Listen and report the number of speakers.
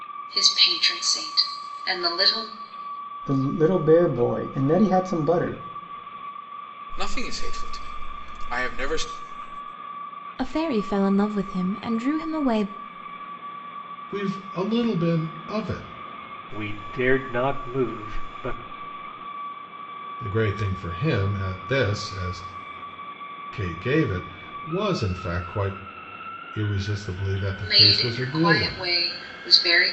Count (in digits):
6